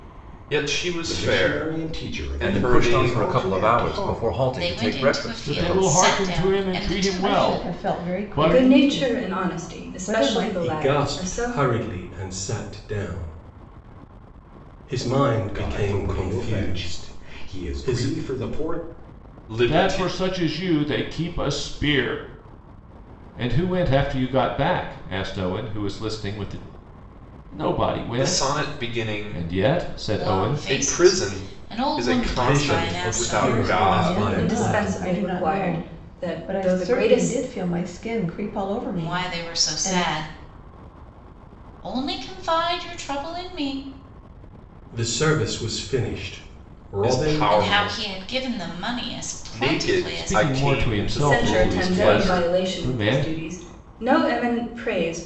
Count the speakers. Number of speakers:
eight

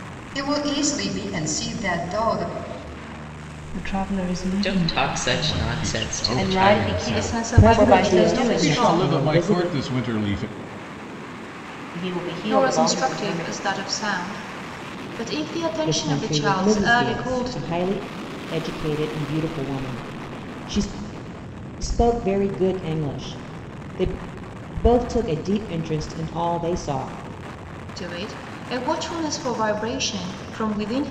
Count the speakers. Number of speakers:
seven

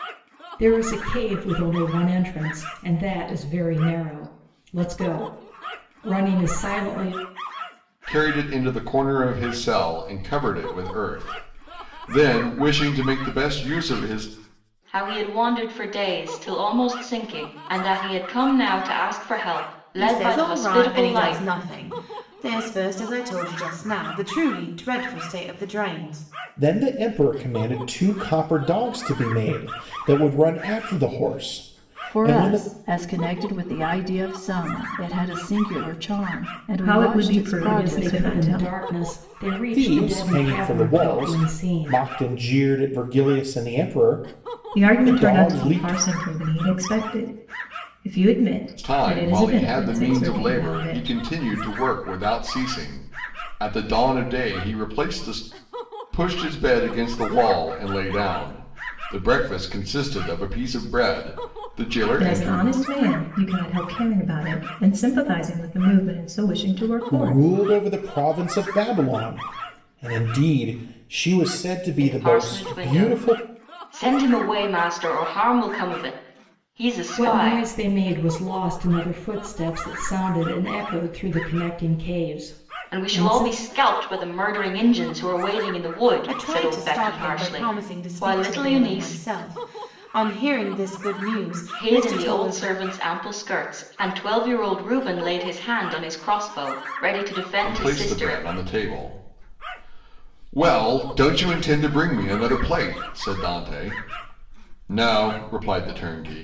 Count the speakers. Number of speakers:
seven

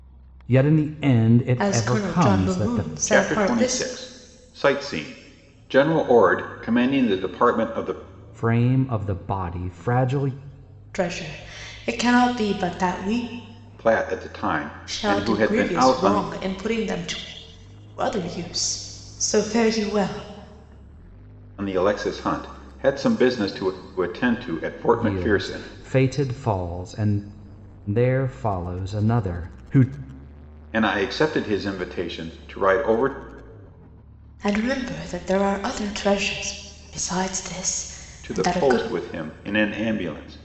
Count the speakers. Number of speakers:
three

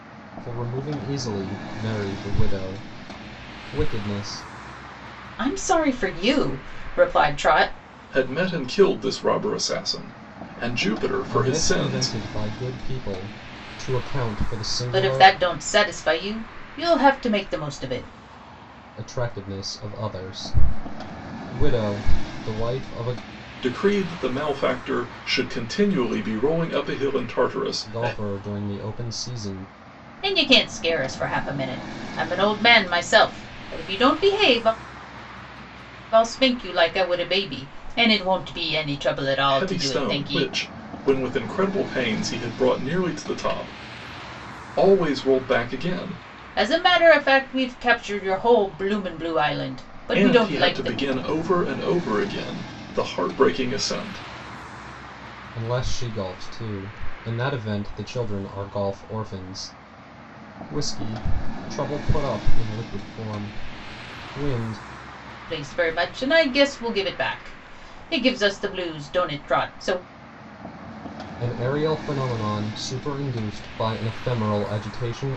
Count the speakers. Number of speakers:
three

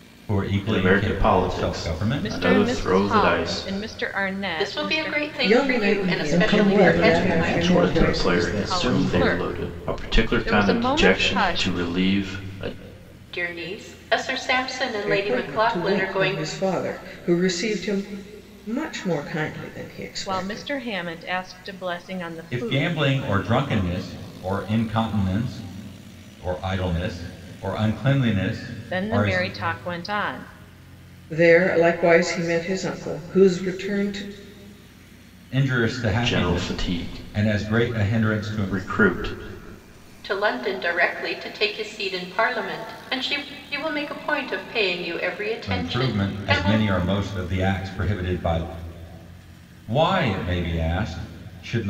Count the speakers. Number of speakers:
six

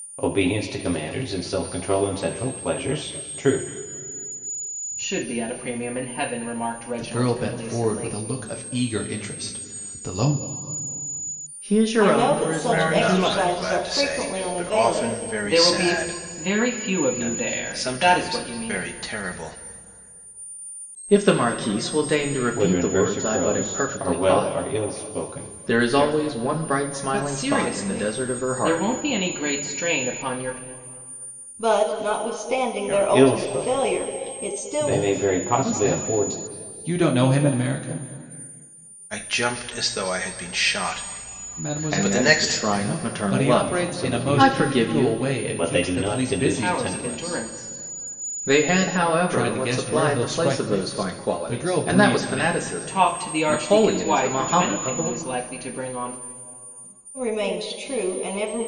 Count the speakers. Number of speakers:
six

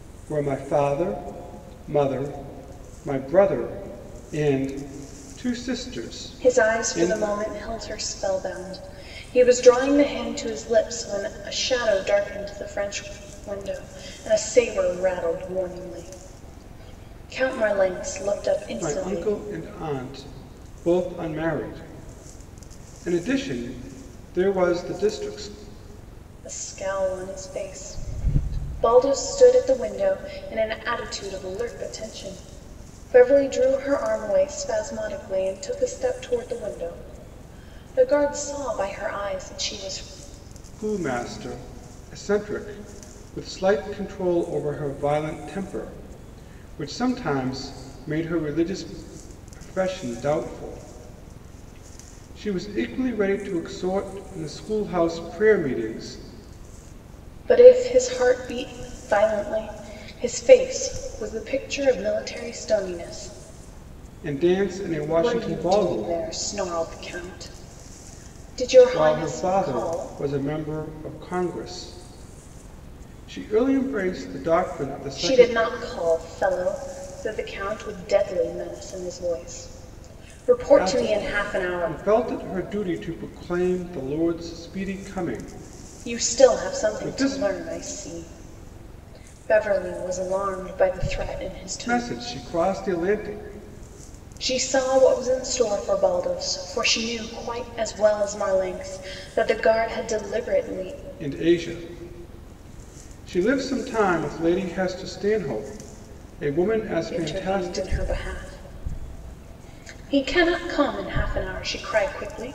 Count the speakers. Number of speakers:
two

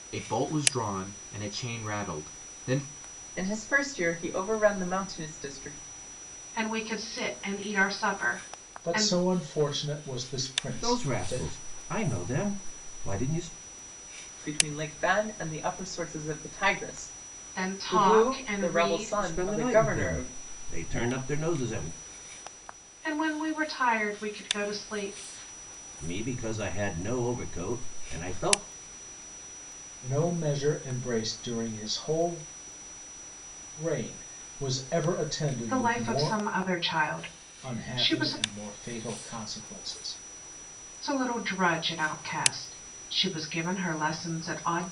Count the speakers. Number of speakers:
five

